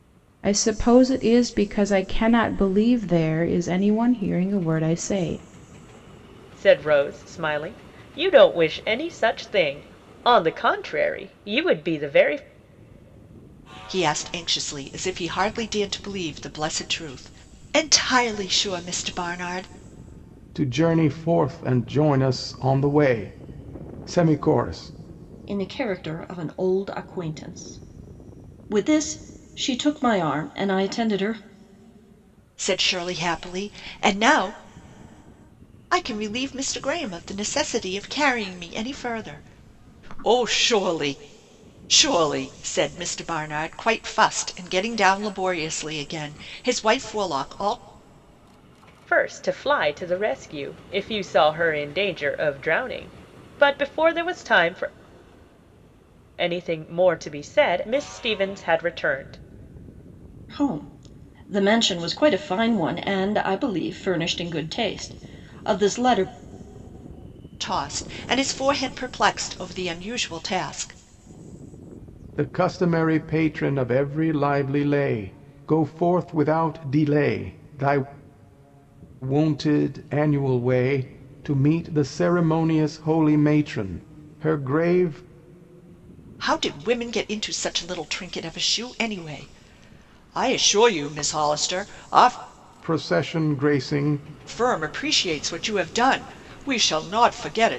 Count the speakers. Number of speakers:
five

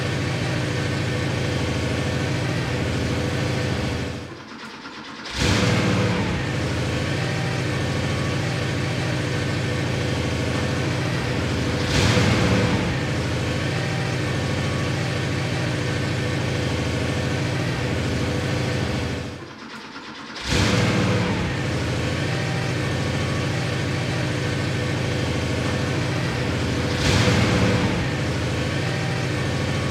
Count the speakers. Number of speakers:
zero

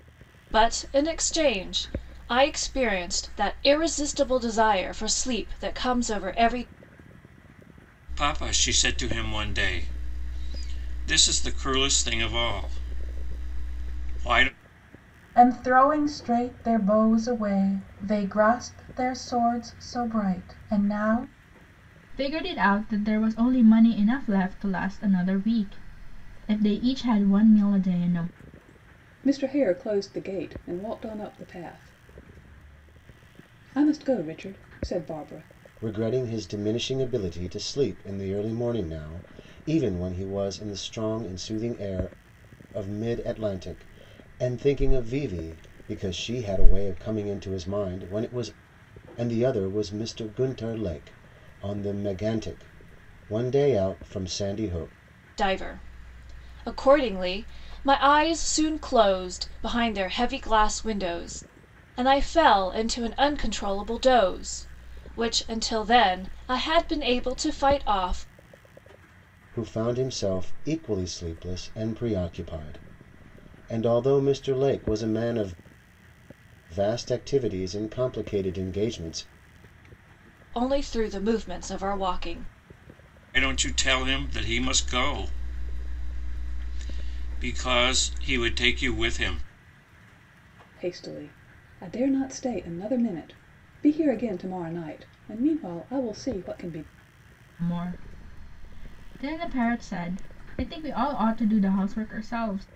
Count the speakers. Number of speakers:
six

